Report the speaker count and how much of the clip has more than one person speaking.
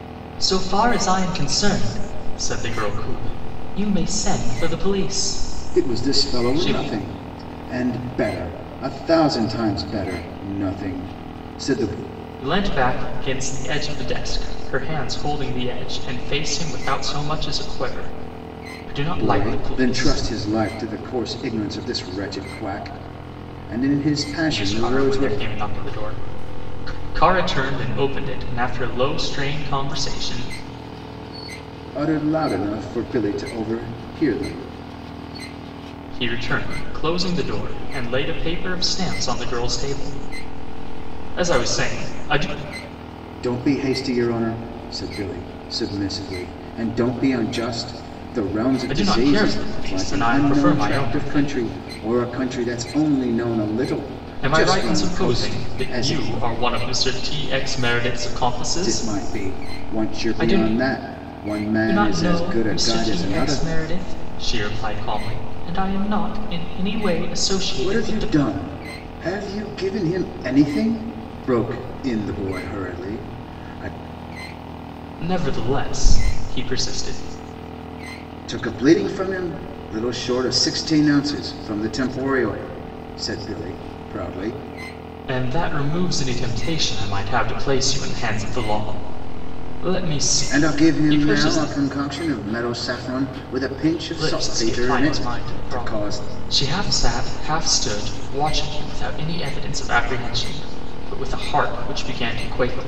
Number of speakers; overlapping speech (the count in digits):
2, about 14%